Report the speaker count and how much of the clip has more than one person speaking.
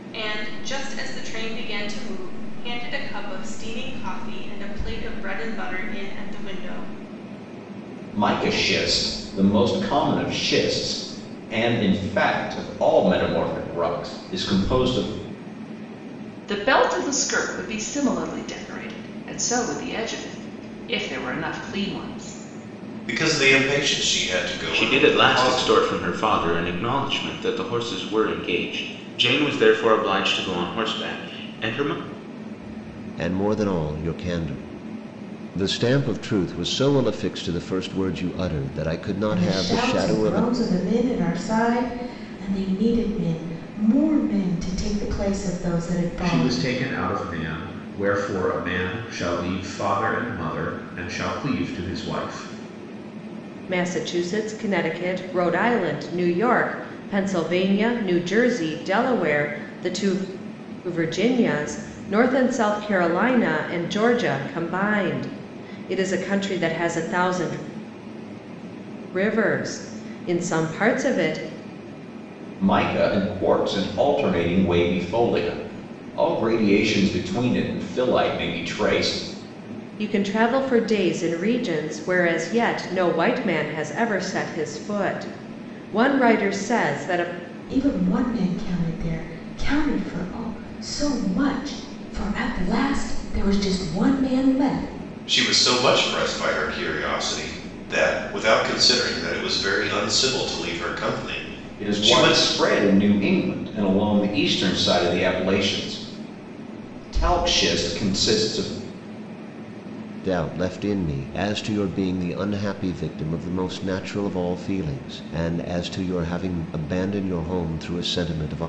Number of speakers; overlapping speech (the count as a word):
nine, about 3%